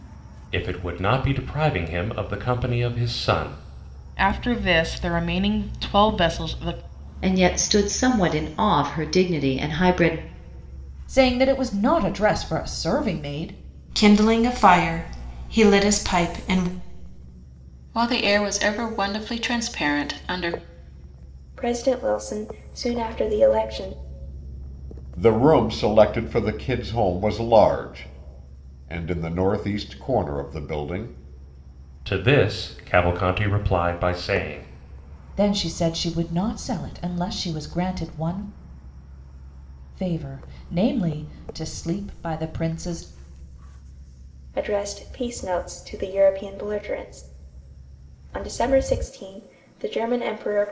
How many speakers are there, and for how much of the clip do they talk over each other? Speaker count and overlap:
eight, no overlap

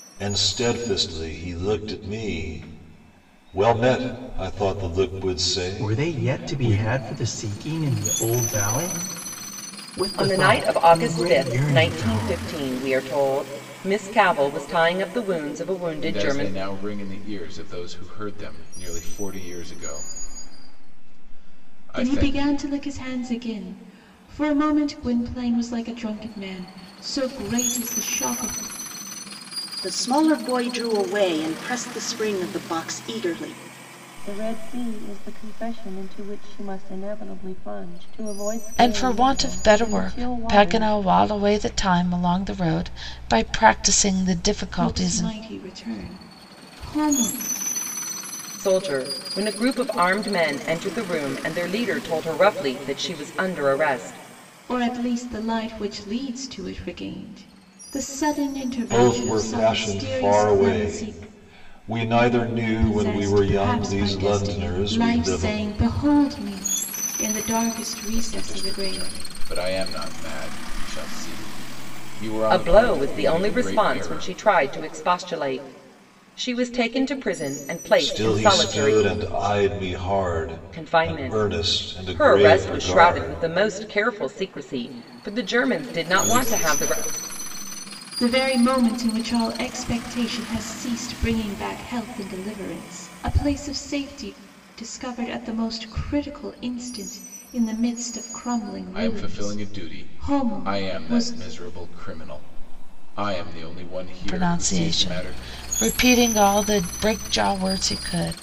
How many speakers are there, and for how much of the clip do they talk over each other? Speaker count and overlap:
eight, about 22%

